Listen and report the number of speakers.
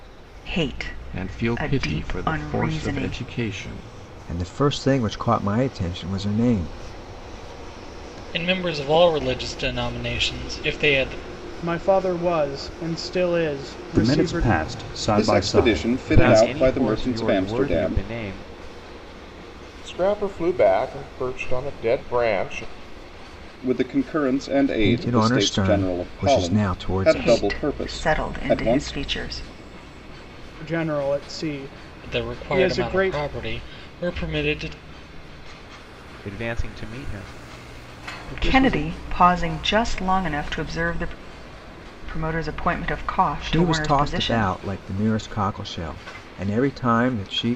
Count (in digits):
9